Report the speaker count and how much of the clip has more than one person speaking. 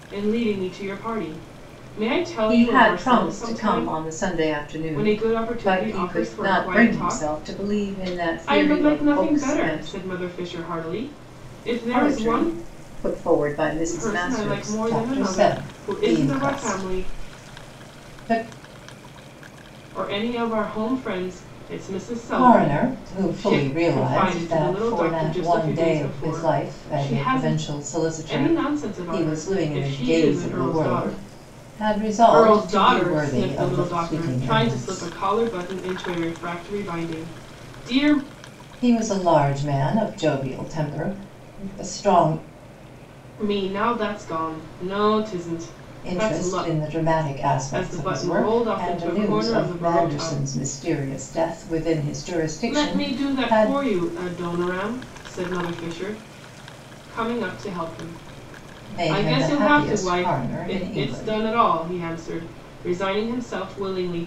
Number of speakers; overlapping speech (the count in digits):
2, about 45%